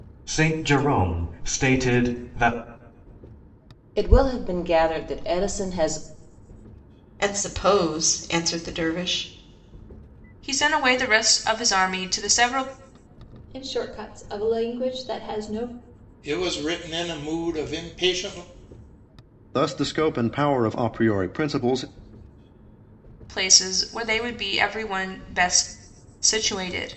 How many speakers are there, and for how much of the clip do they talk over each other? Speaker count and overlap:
7, no overlap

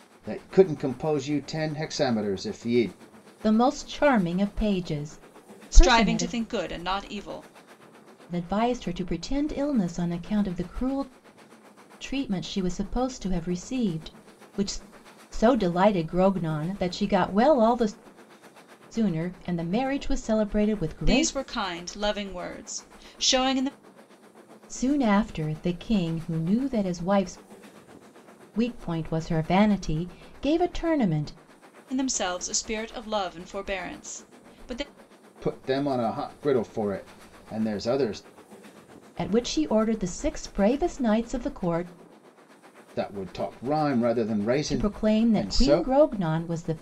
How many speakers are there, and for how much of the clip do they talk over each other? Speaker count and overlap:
3, about 5%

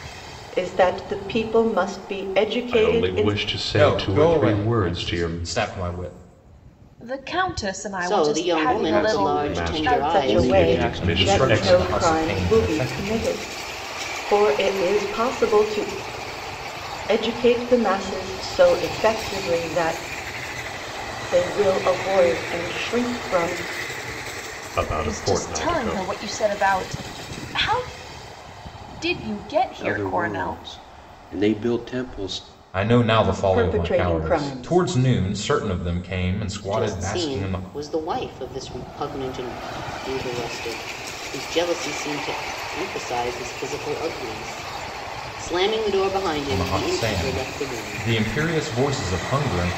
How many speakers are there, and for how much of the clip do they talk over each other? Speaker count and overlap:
6, about 27%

